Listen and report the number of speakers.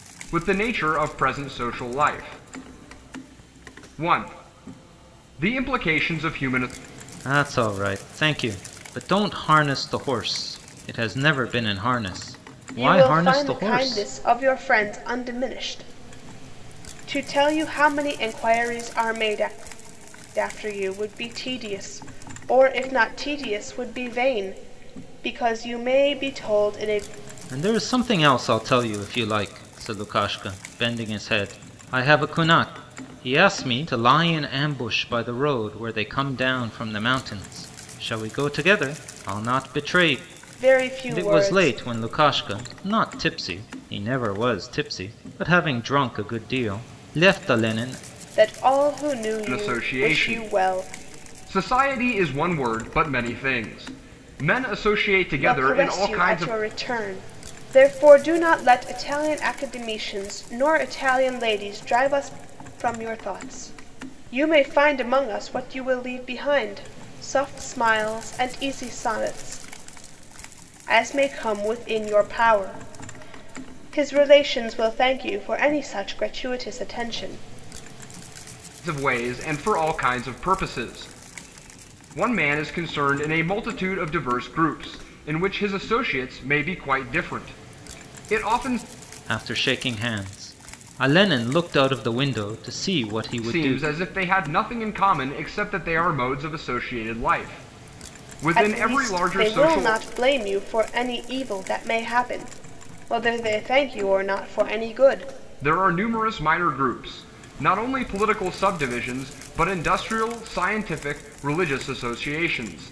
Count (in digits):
3